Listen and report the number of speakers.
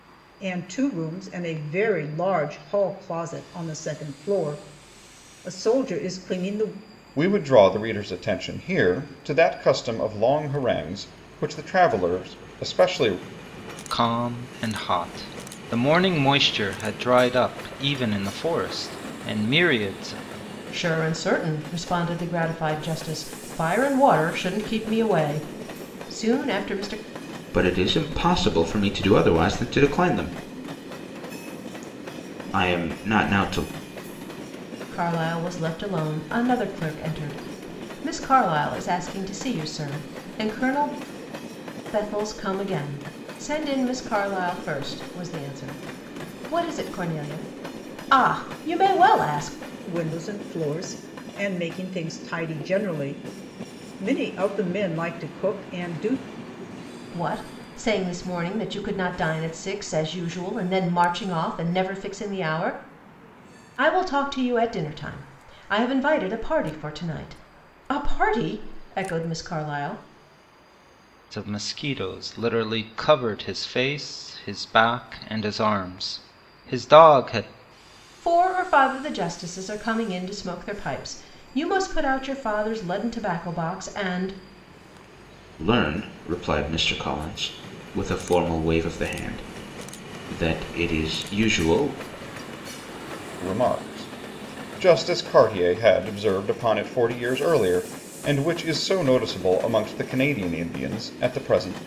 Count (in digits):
5